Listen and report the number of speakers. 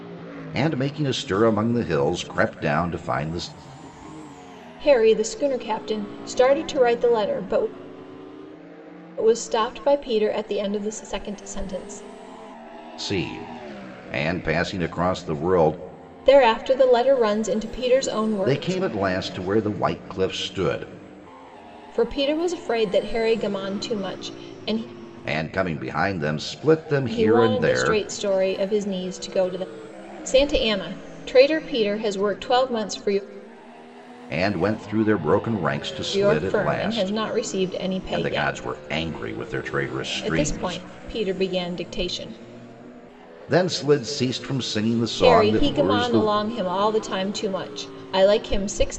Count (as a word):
two